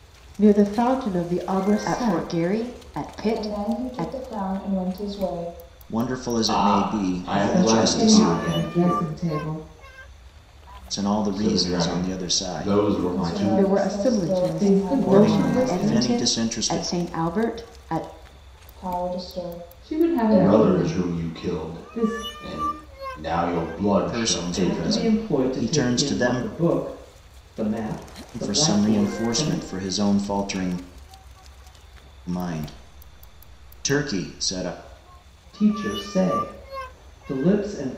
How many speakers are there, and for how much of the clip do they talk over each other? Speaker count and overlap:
seven, about 41%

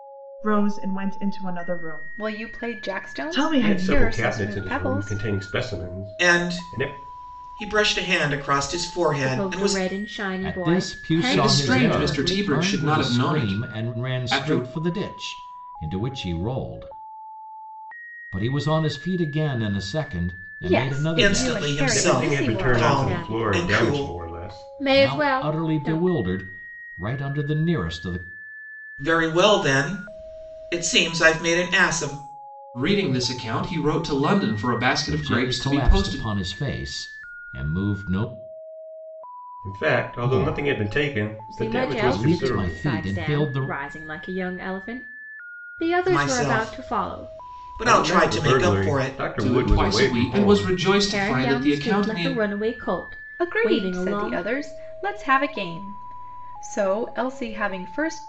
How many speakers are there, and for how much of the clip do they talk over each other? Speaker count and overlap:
seven, about 43%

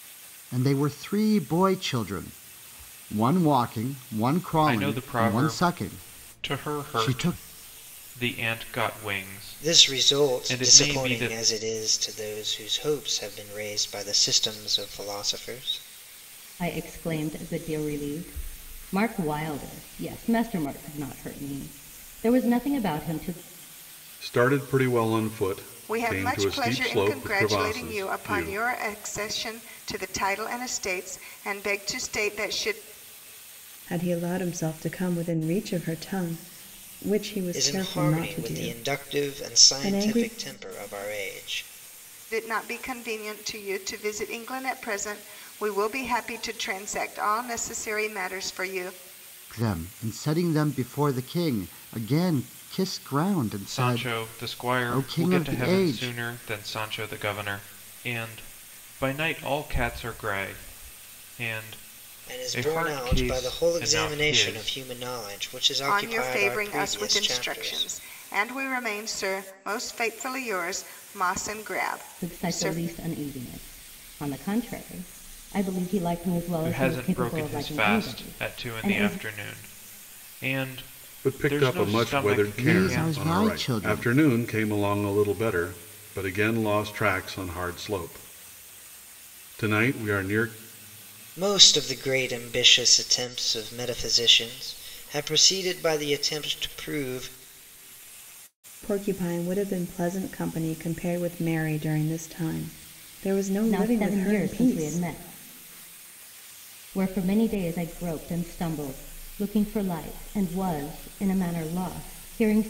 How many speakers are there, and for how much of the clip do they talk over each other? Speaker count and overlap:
seven, about 22%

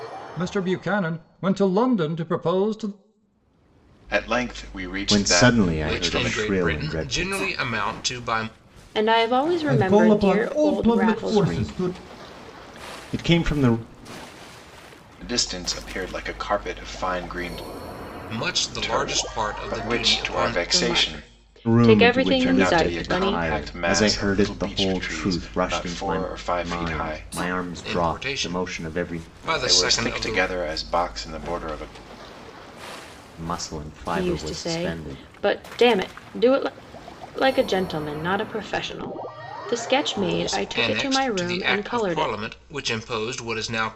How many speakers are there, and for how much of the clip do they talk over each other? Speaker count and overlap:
six, about 41%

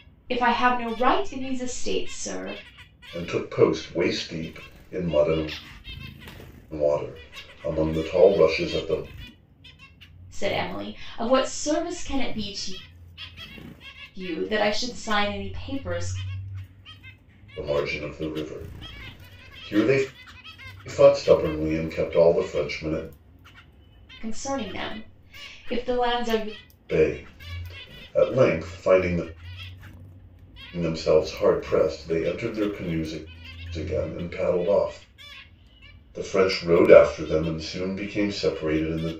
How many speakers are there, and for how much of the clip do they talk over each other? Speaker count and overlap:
two, no overlap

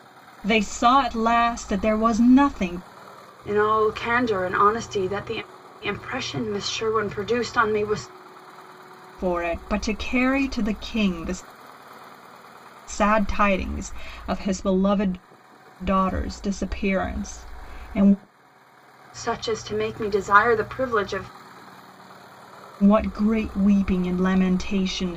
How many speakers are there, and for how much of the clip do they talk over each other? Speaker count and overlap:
two, no overlap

